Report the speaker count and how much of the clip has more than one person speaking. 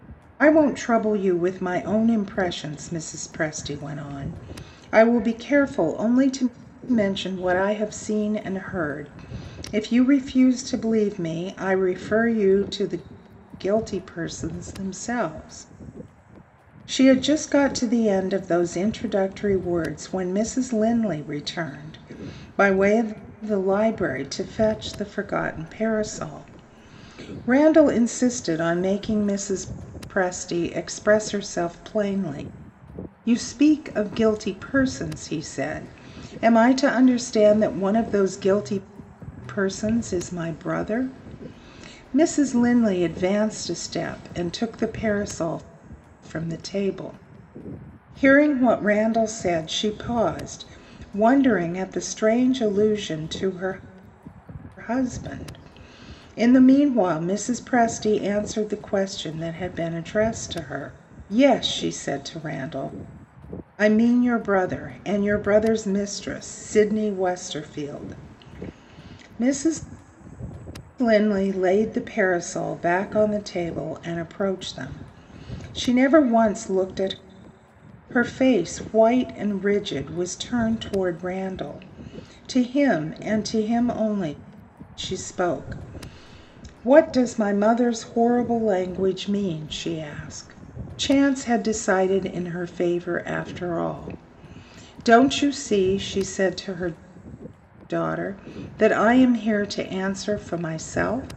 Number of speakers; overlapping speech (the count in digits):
1, no overlap